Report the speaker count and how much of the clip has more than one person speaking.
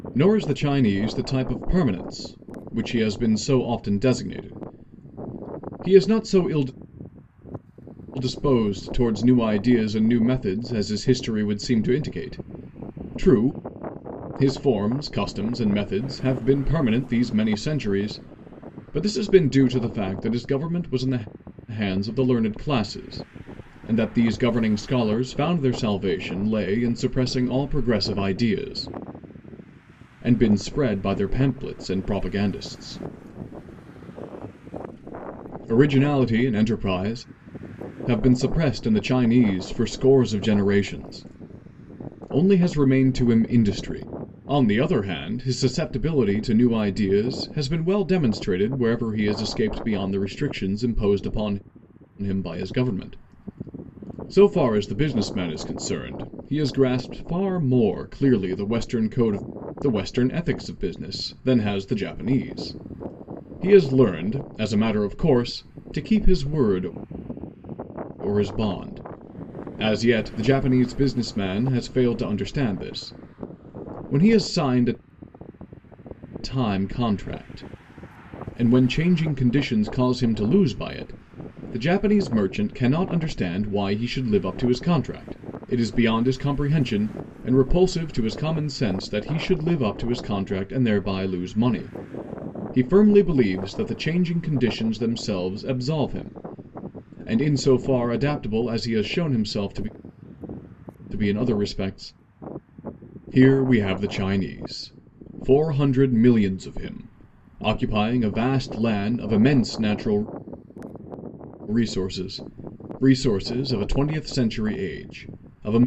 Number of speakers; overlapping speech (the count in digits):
1, no overlap